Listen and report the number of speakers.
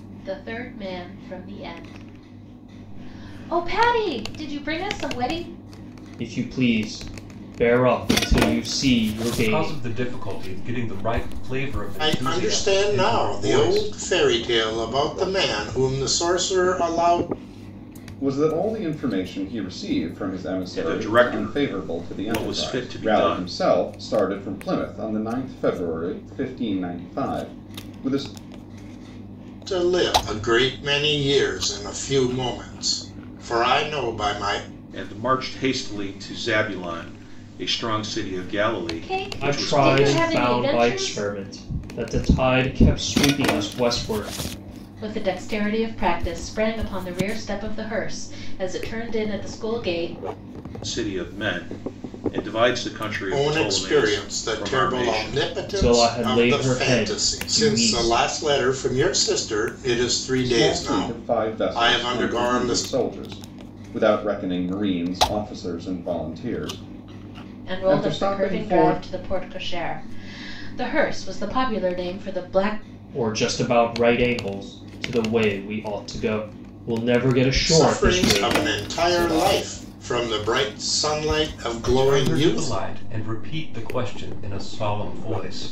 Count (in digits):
6